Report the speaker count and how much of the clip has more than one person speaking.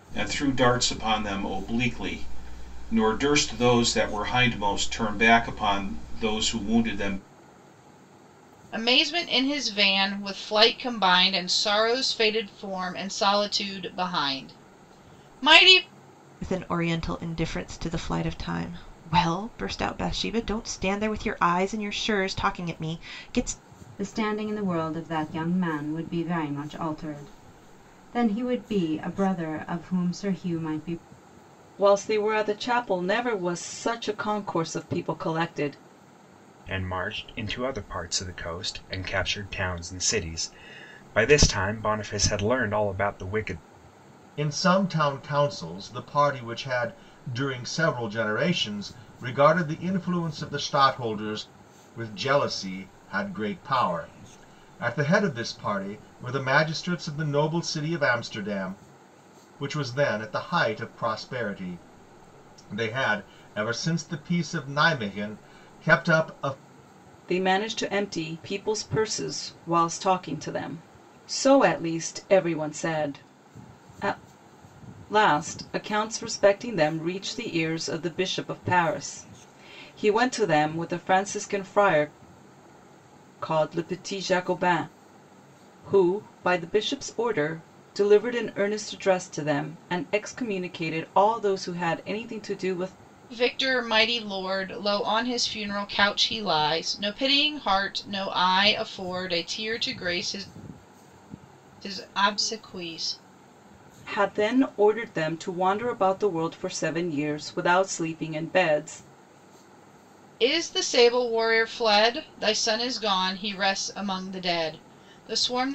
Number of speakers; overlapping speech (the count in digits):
7, no overlap